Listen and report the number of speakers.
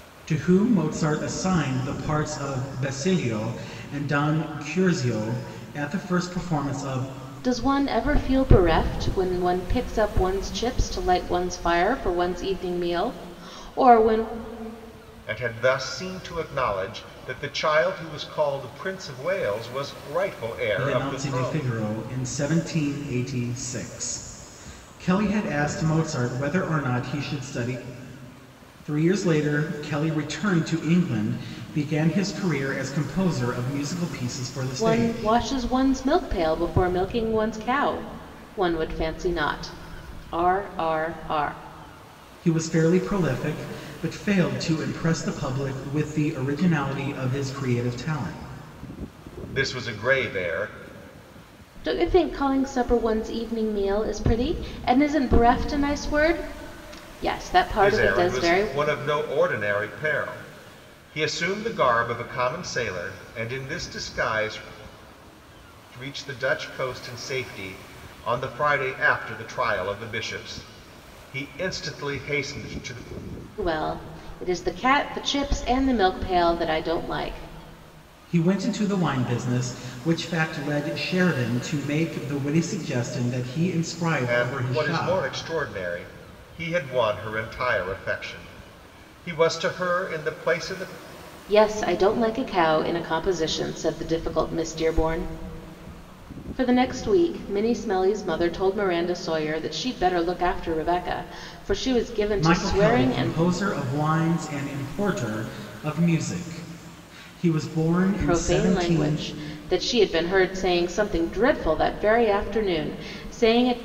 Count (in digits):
3